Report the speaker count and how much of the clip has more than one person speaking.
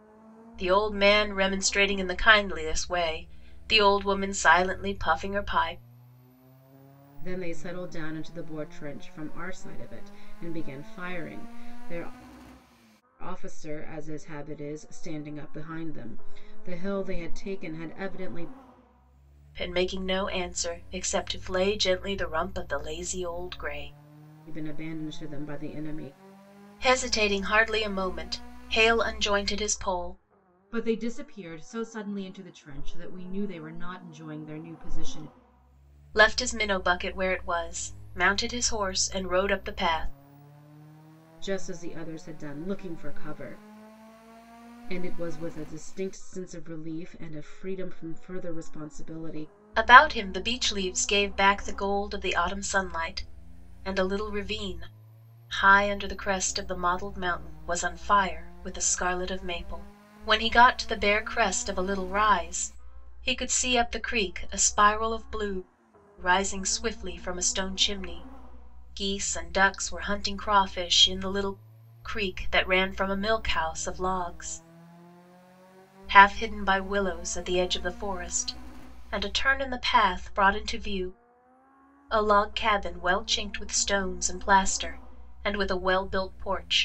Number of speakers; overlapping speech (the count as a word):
two, no overlap